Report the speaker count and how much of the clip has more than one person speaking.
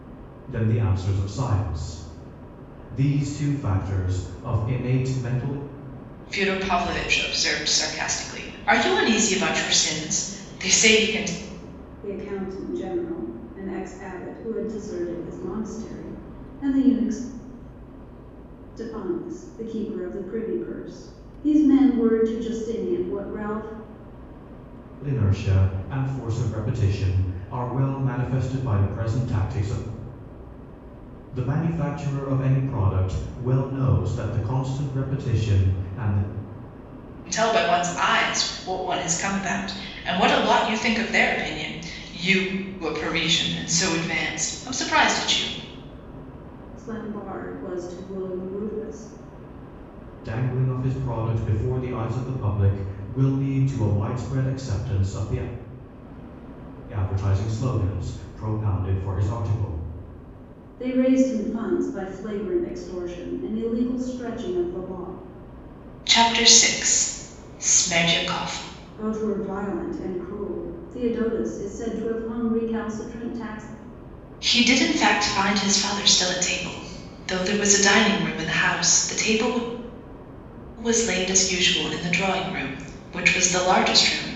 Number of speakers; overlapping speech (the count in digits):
3, no overlap